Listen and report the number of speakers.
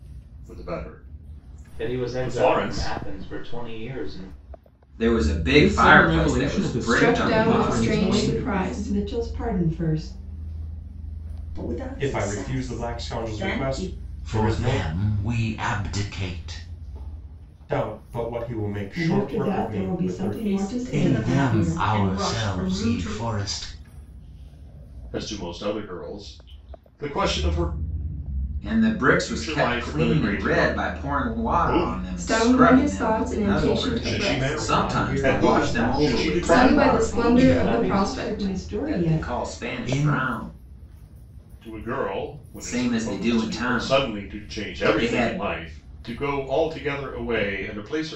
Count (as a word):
nine